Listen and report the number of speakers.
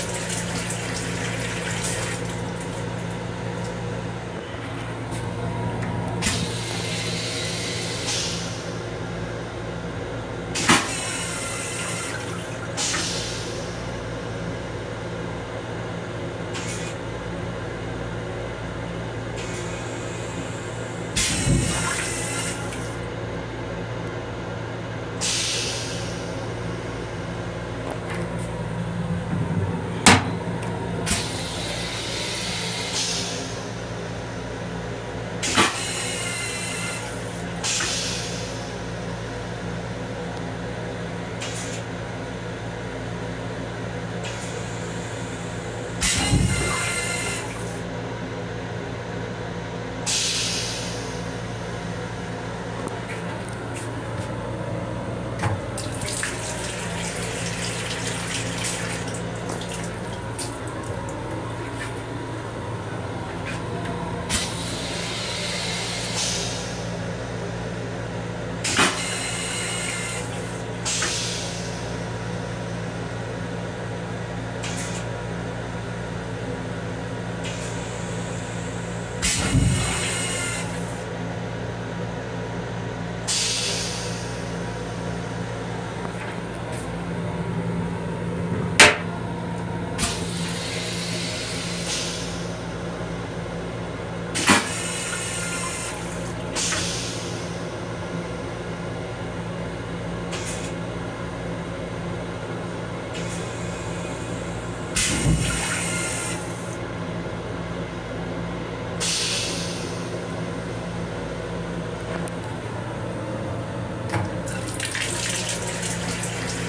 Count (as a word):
zero